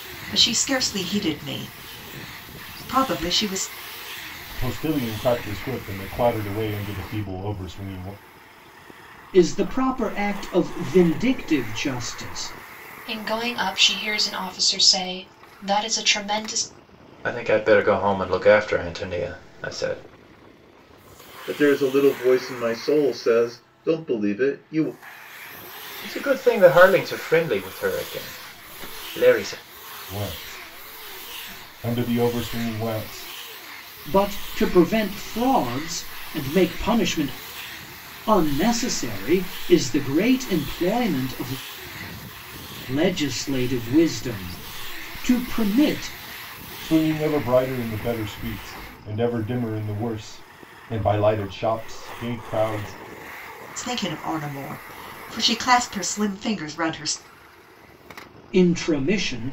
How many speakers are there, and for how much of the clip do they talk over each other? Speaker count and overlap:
6, no overlap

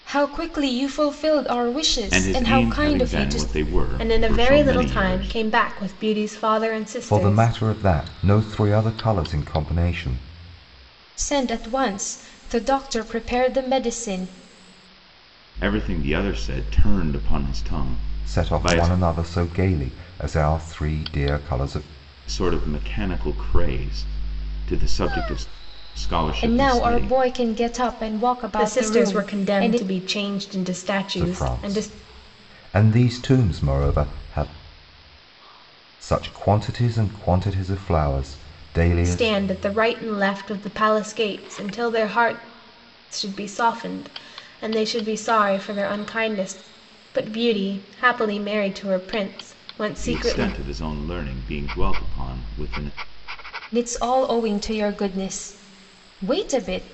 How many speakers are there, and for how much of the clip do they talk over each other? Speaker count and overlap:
4, about 14%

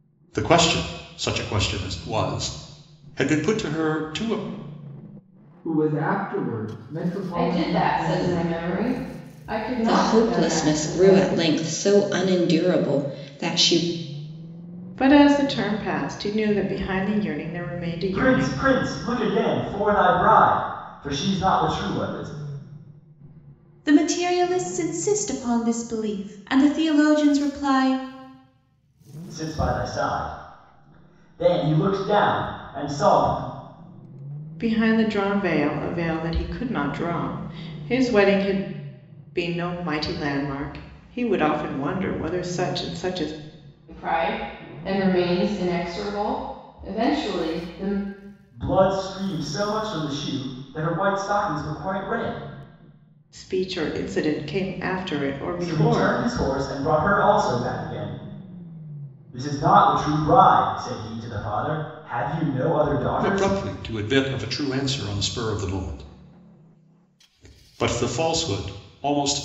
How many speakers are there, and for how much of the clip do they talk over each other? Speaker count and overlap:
7, about 6%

